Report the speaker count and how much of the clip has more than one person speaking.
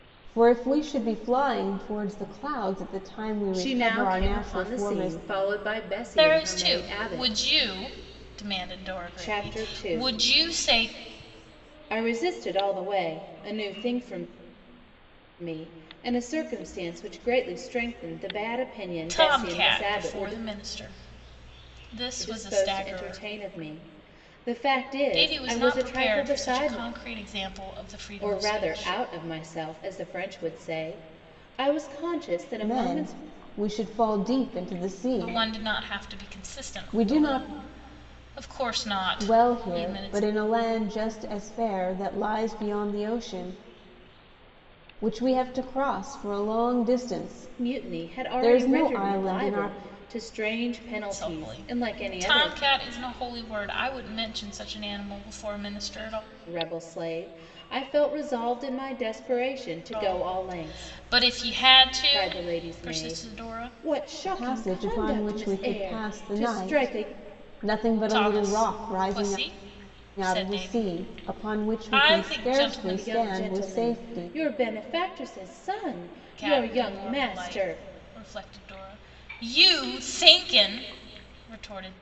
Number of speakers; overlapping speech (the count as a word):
three, about 37%